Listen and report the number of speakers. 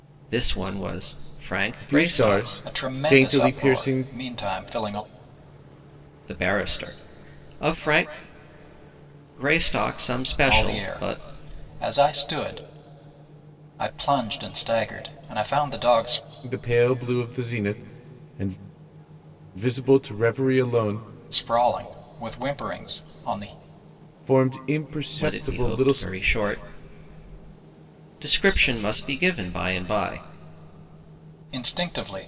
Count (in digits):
3